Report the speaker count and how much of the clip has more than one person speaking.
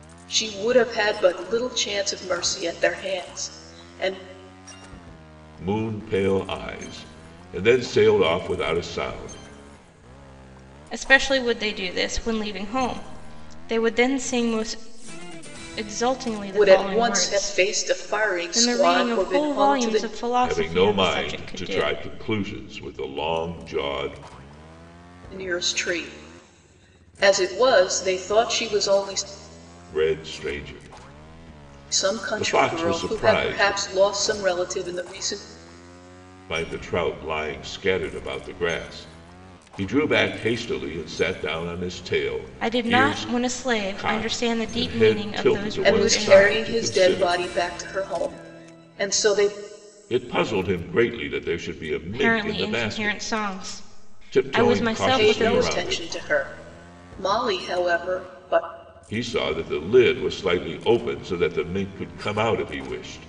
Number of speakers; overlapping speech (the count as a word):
three, about 21%